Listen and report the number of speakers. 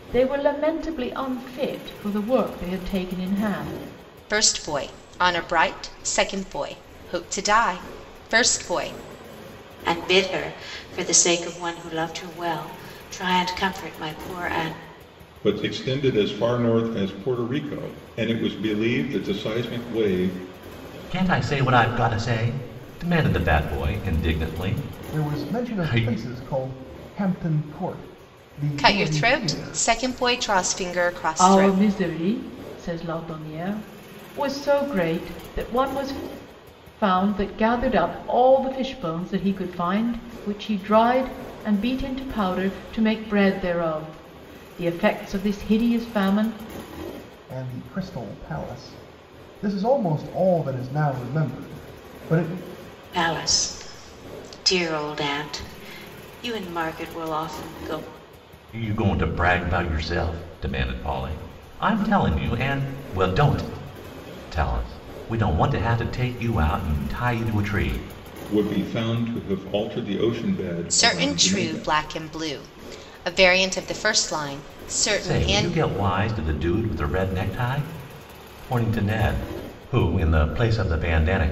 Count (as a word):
six